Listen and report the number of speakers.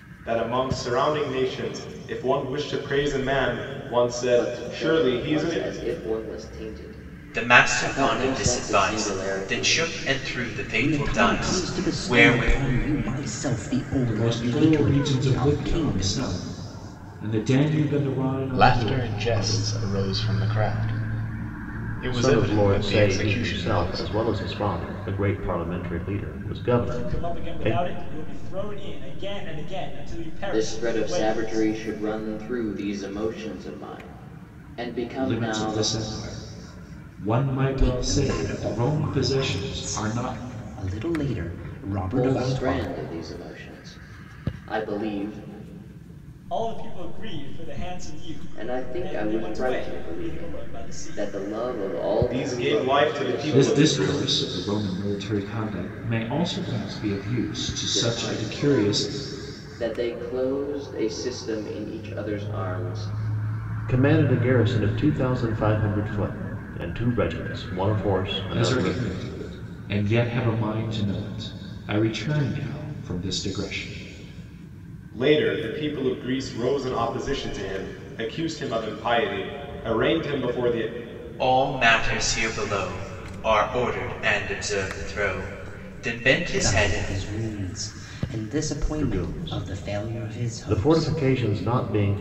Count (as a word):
eight